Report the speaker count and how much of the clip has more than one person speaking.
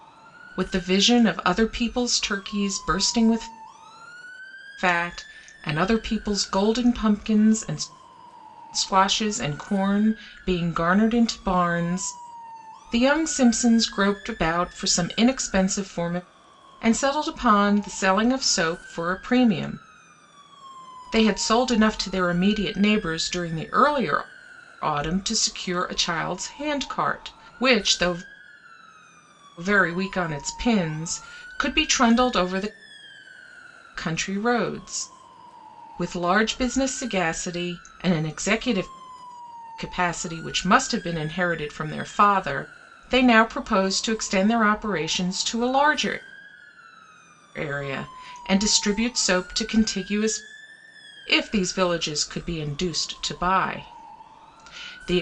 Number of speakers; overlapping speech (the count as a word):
one, no overlap